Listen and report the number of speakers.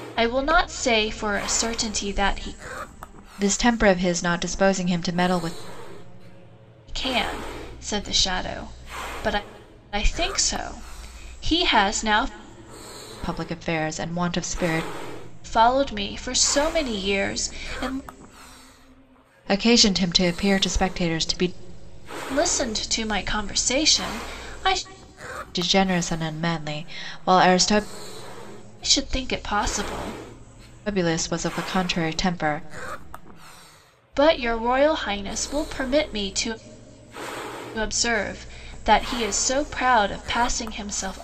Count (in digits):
2